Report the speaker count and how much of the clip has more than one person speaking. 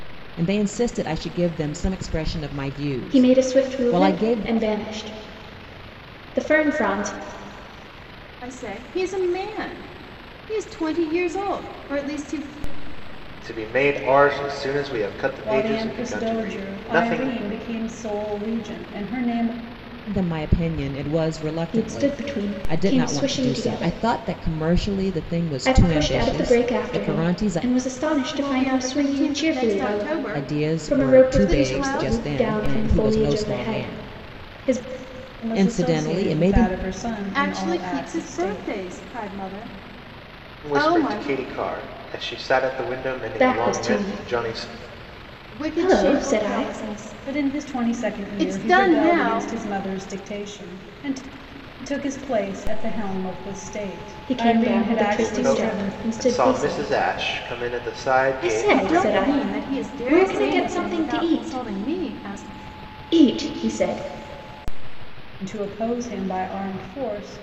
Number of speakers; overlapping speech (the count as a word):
five, about 44%